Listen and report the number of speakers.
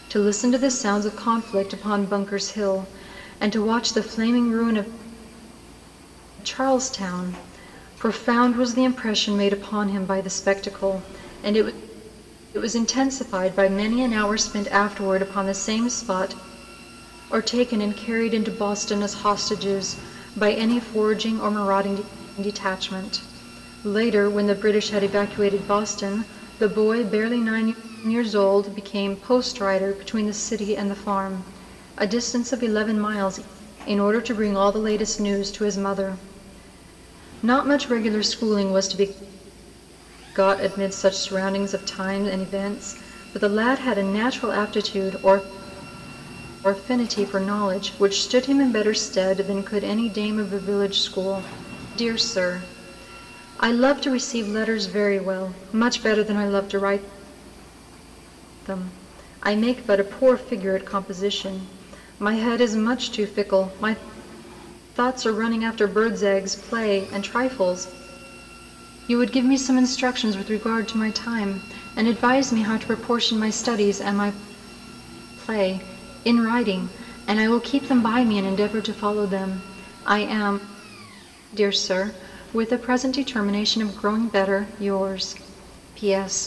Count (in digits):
1